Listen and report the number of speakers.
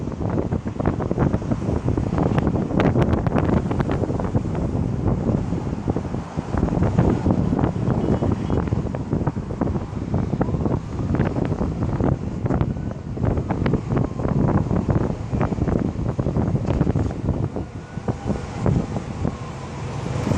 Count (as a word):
zero